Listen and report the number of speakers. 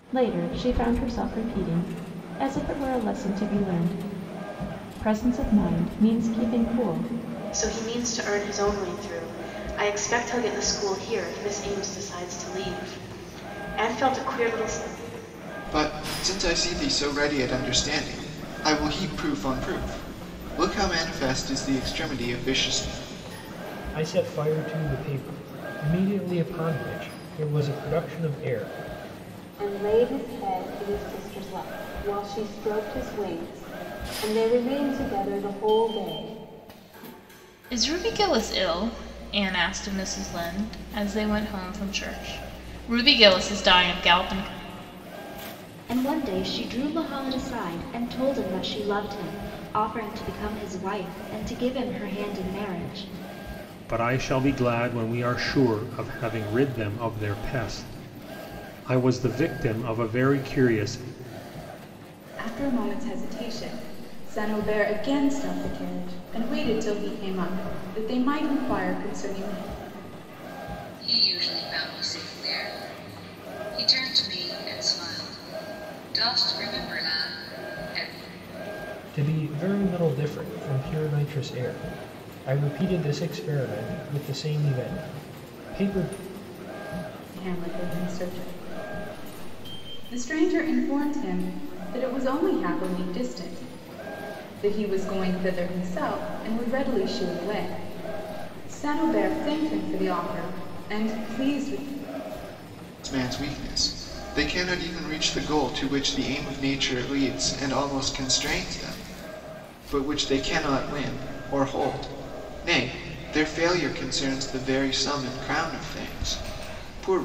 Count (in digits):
10